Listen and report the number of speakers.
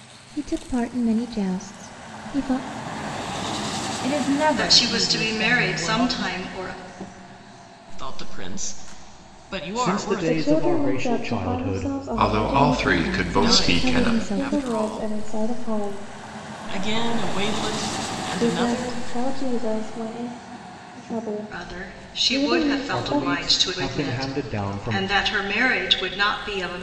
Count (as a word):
seven